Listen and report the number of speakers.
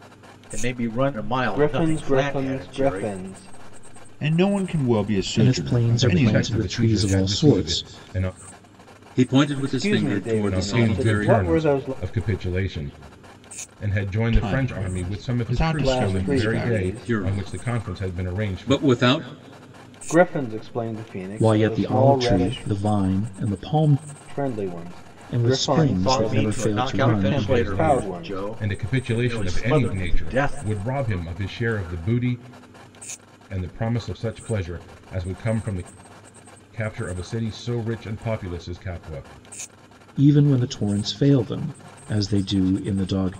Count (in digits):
6